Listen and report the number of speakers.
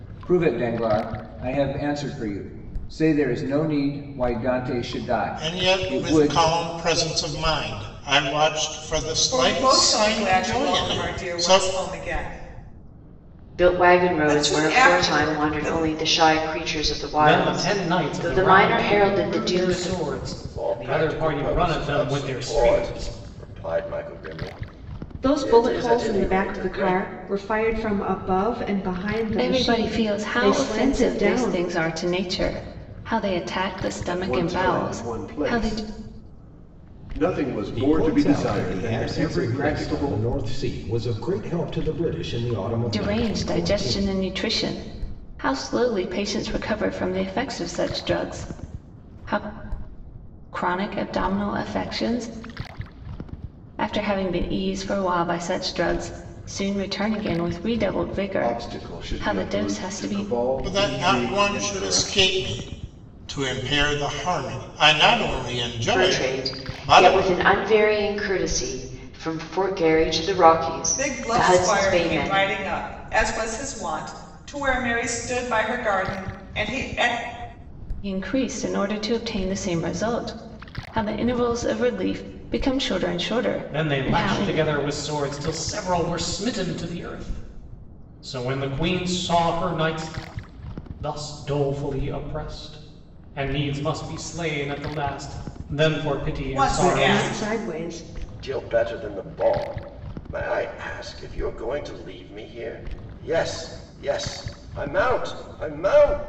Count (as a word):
ten